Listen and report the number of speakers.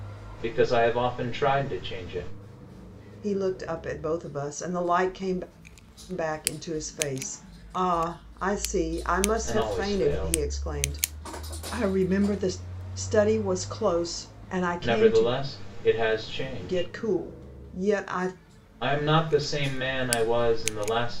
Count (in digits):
2